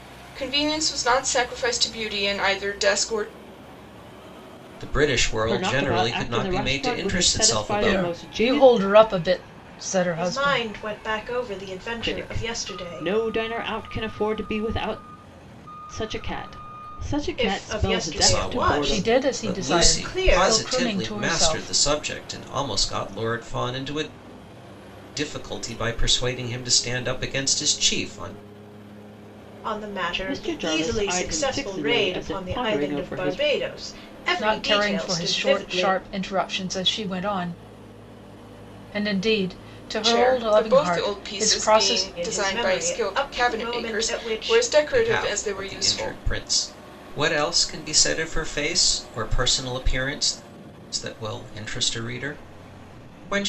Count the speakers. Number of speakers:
5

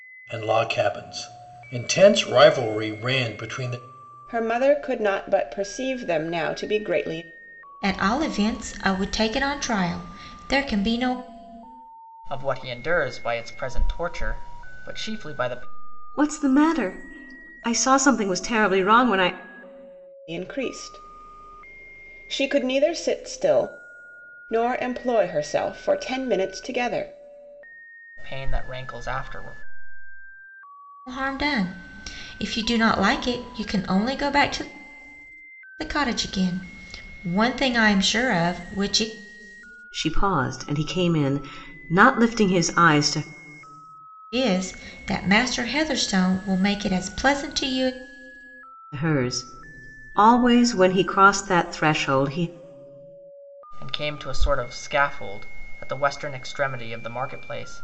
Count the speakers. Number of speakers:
5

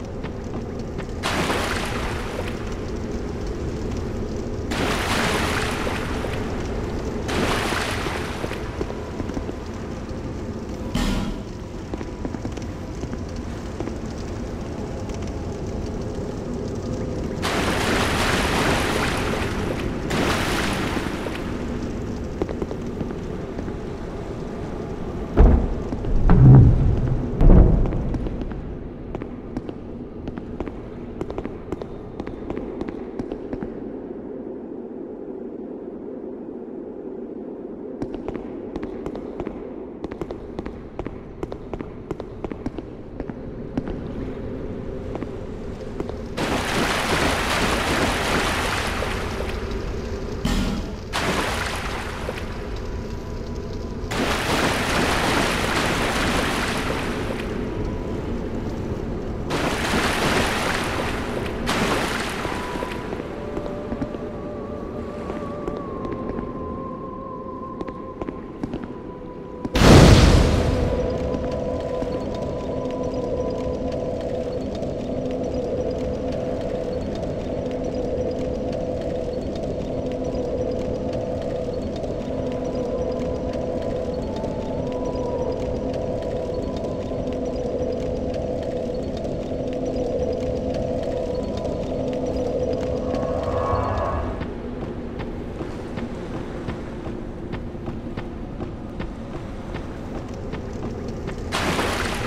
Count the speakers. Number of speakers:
0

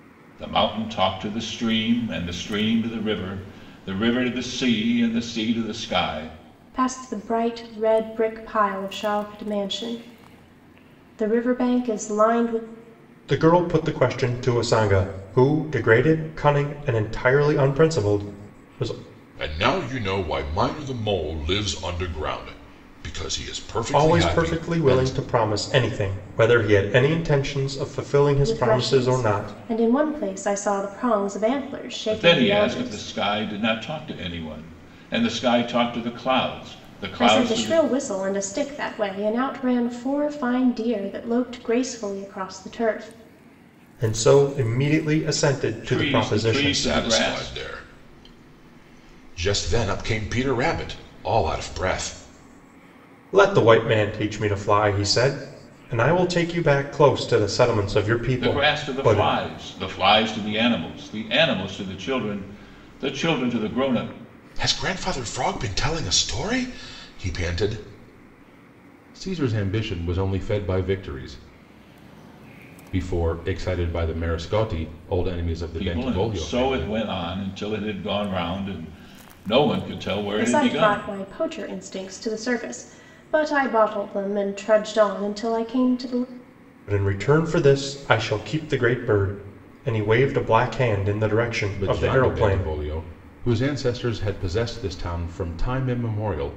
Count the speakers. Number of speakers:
4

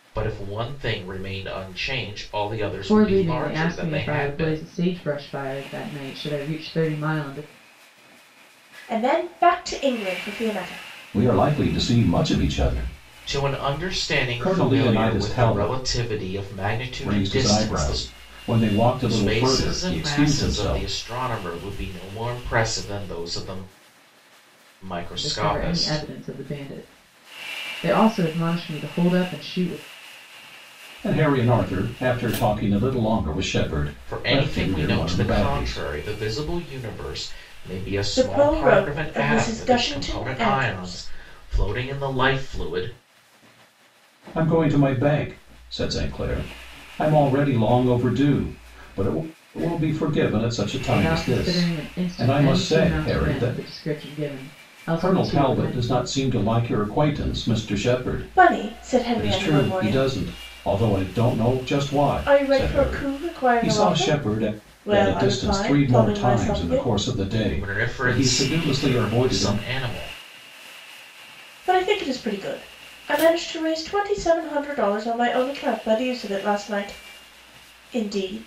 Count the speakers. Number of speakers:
4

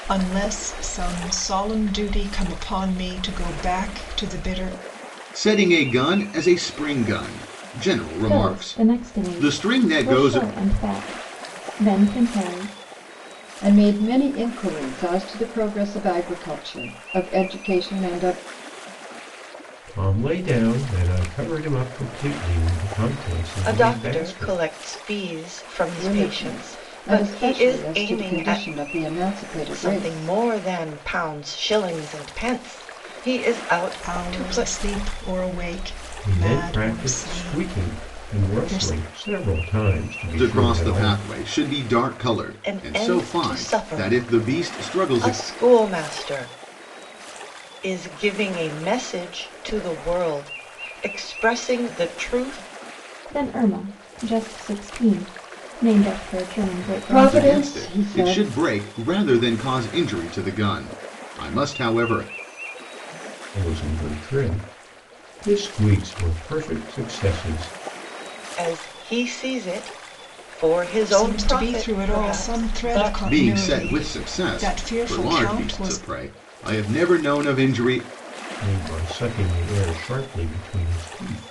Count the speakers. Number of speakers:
6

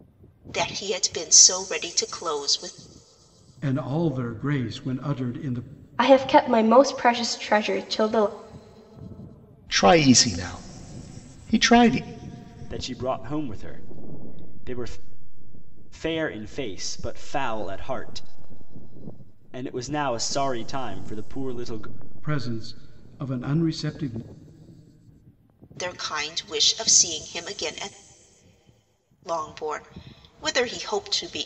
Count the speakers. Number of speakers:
5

